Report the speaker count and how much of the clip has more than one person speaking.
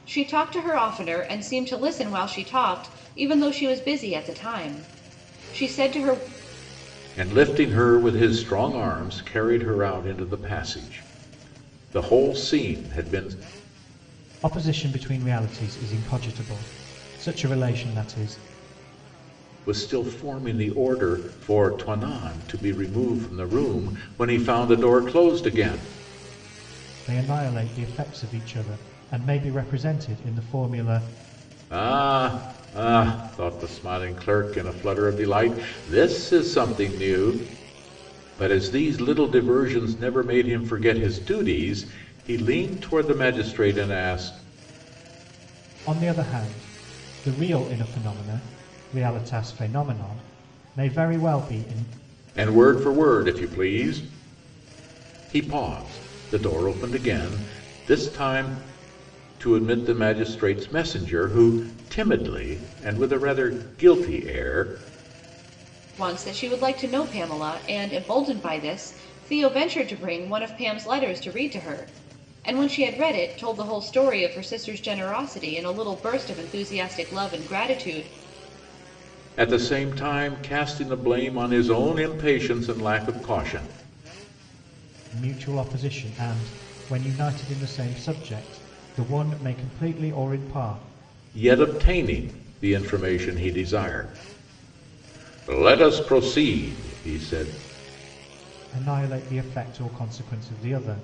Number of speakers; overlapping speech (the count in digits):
3, no overlap